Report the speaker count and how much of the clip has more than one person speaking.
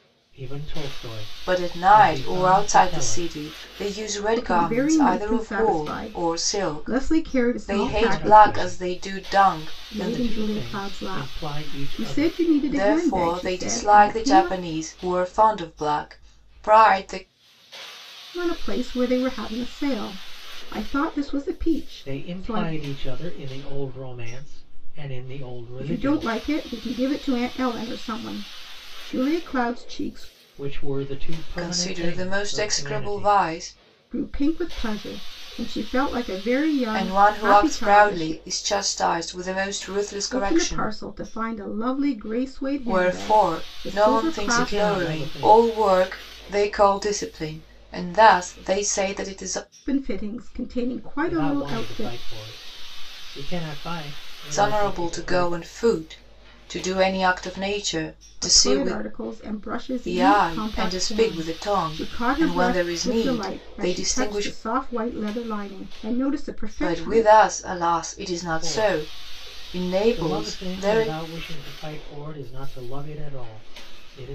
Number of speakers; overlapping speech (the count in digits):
3, about 41%